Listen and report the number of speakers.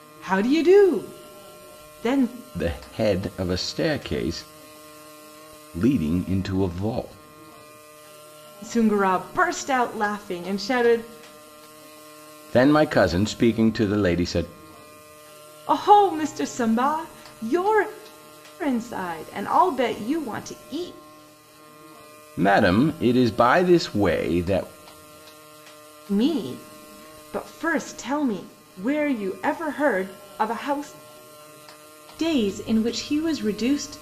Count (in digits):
2